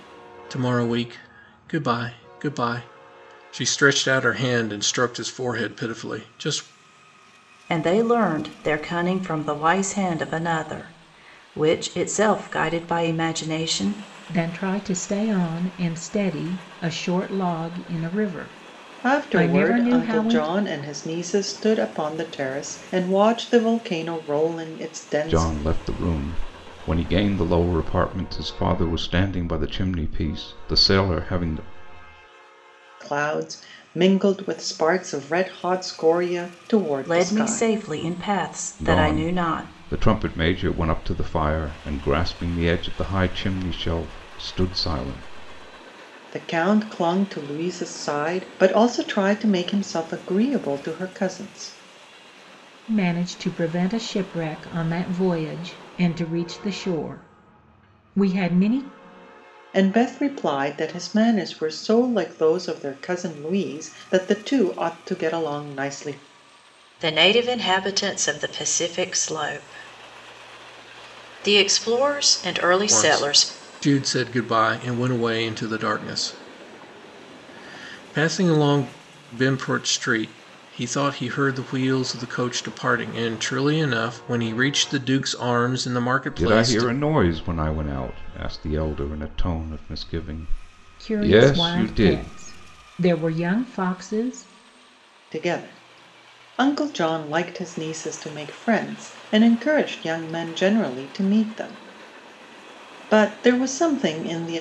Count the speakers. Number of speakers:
5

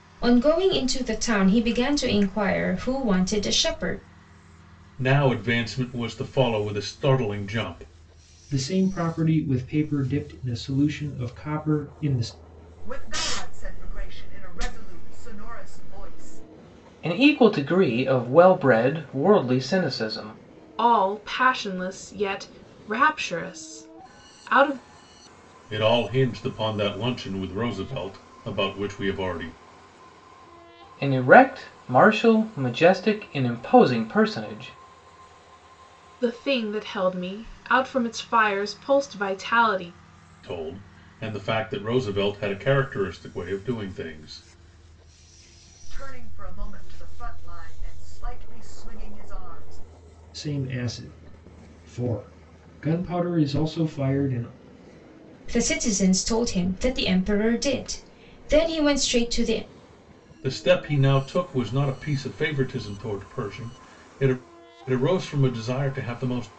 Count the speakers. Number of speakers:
6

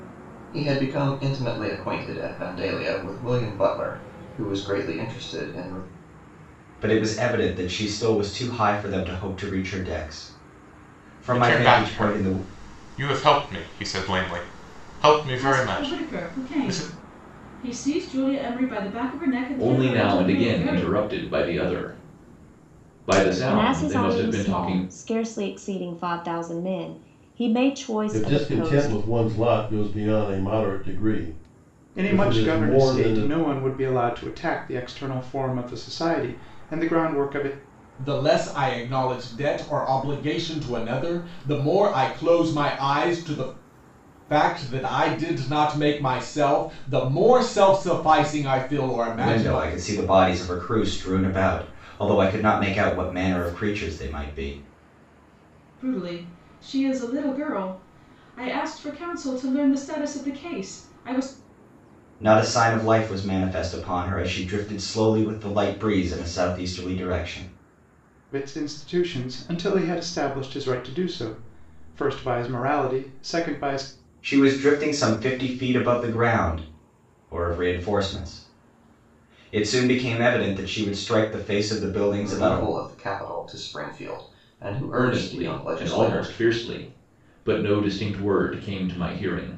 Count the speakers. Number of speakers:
9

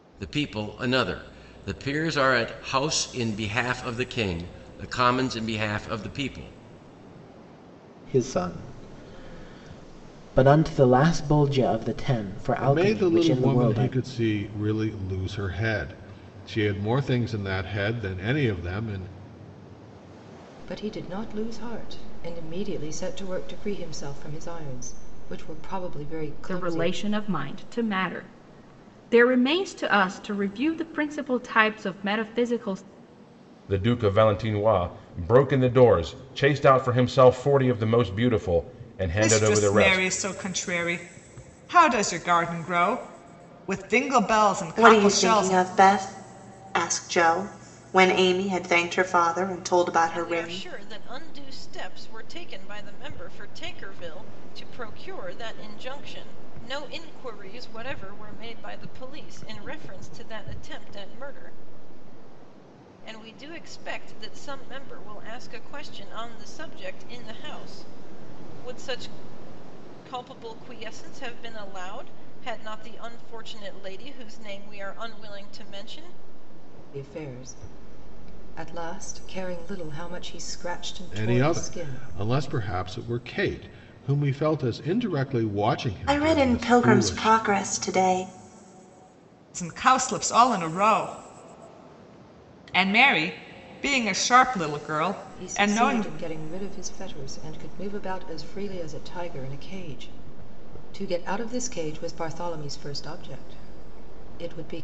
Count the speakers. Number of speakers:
9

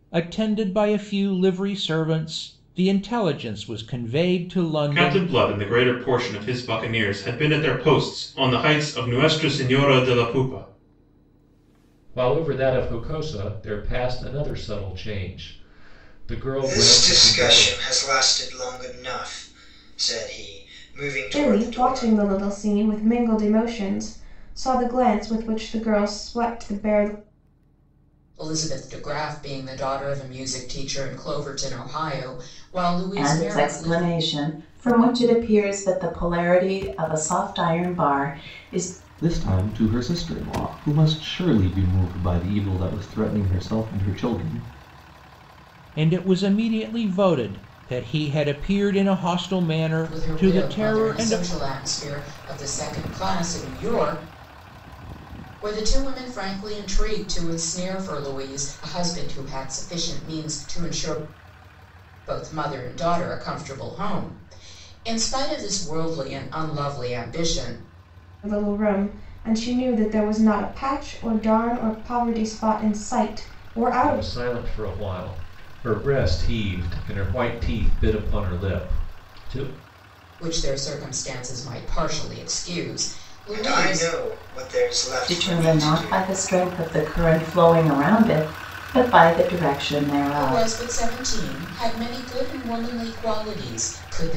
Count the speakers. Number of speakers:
8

